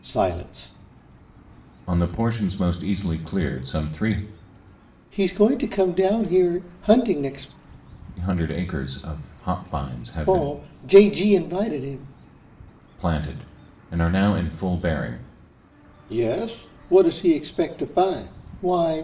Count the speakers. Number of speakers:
two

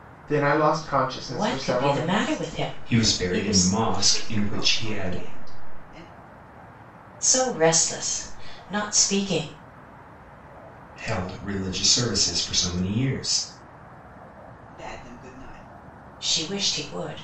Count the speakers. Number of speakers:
four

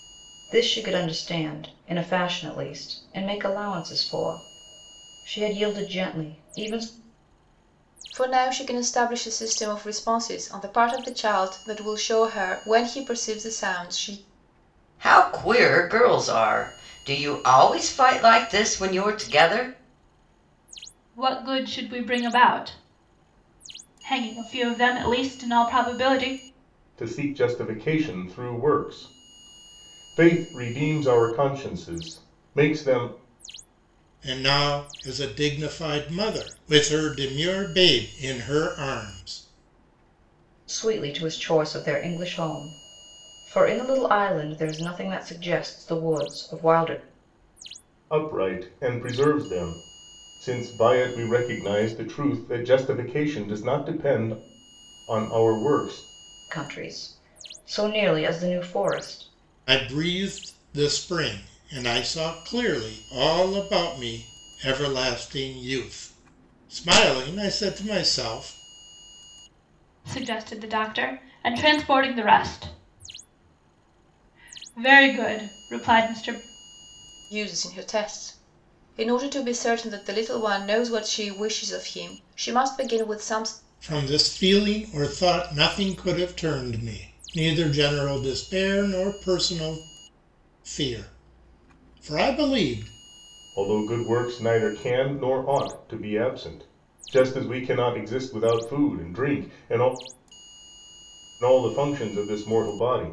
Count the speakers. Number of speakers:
six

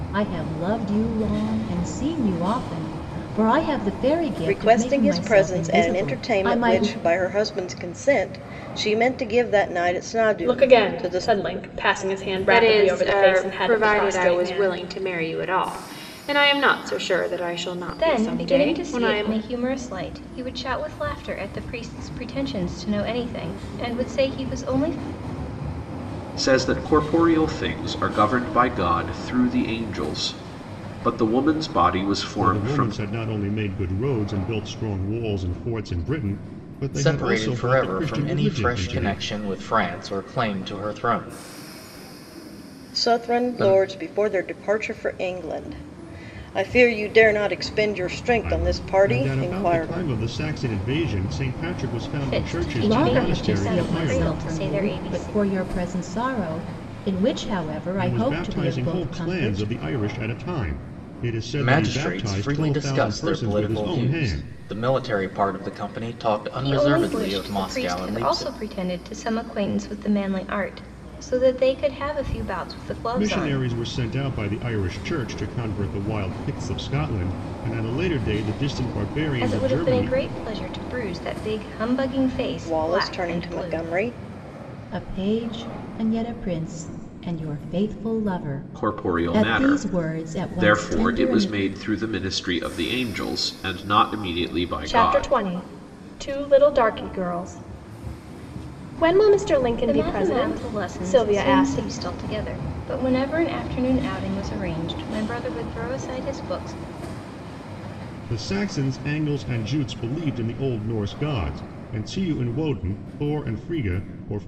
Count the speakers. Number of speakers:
eight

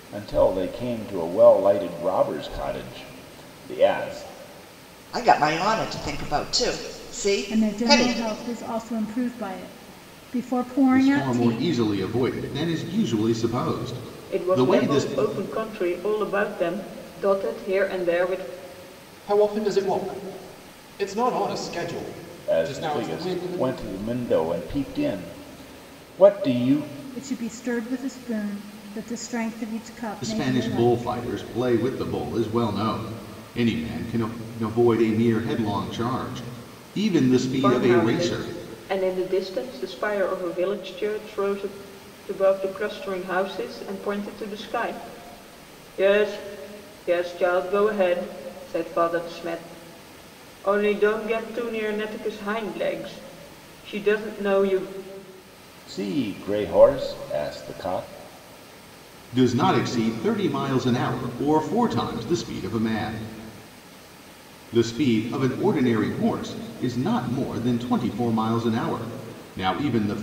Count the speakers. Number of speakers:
six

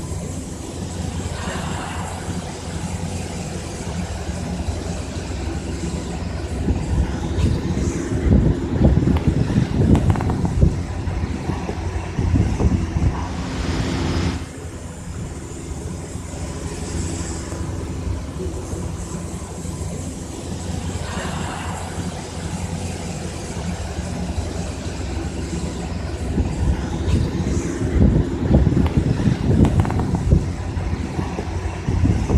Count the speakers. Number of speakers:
zero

